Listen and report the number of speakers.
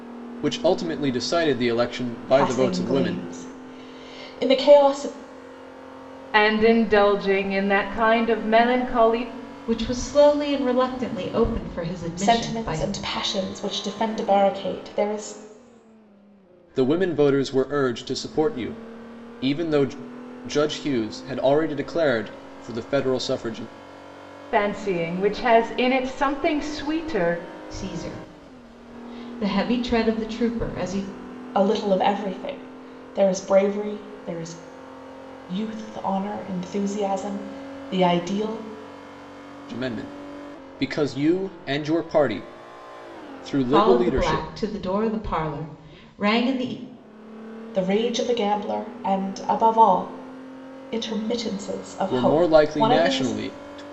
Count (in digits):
4